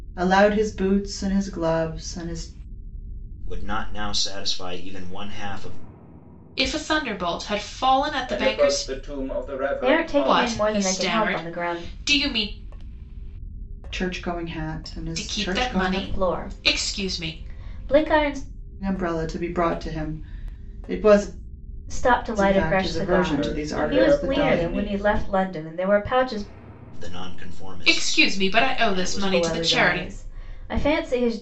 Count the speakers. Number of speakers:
five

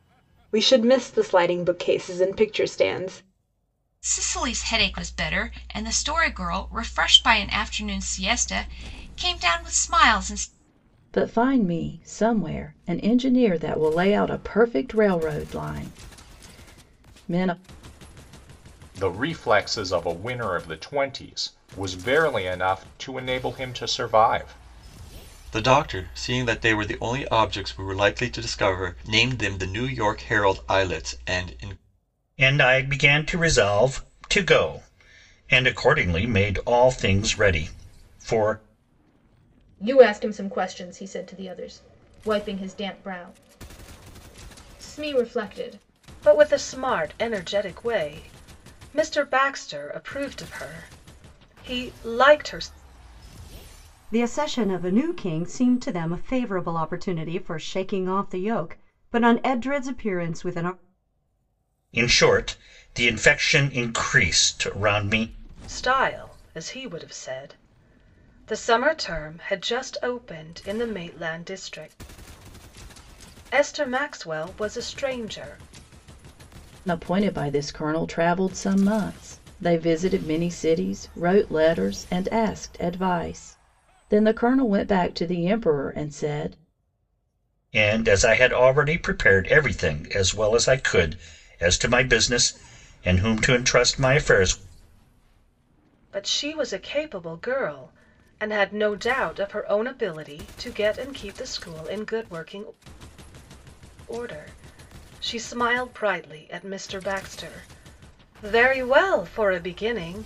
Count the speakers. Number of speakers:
nine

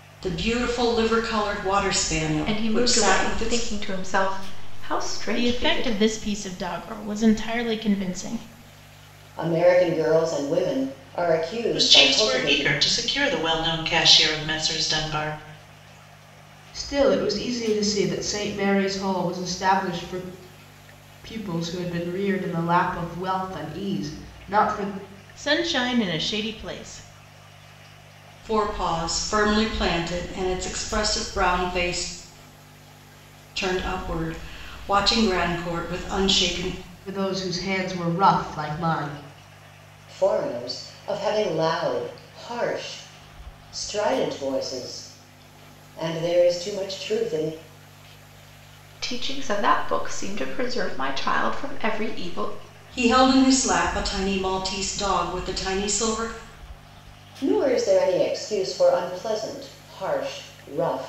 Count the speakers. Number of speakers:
six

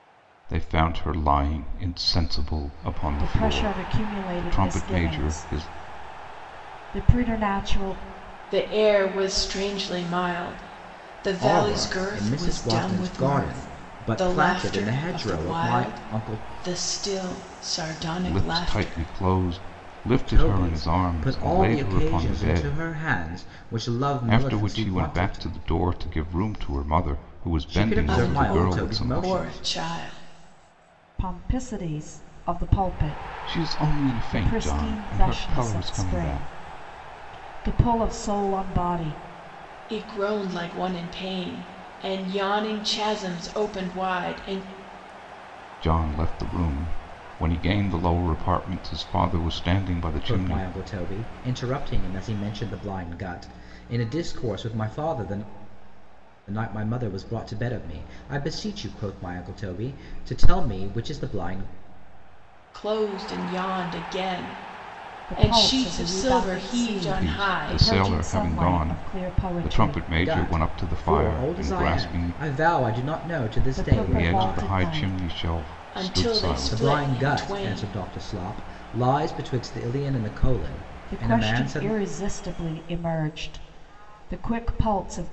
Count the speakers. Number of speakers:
four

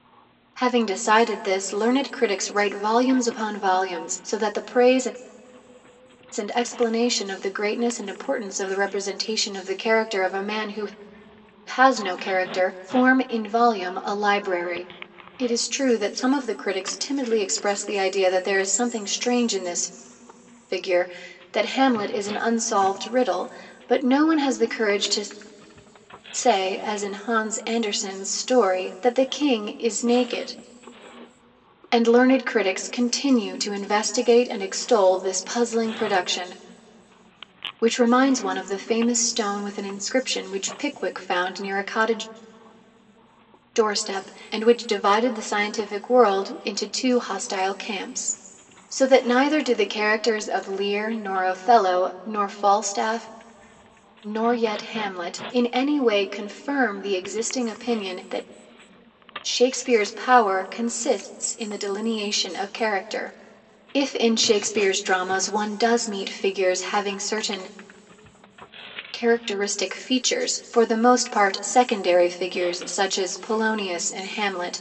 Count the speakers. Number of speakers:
one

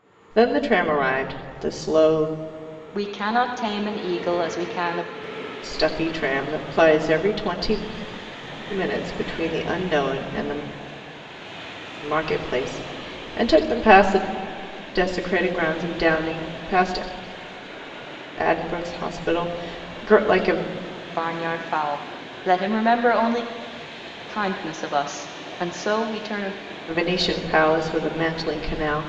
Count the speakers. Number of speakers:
two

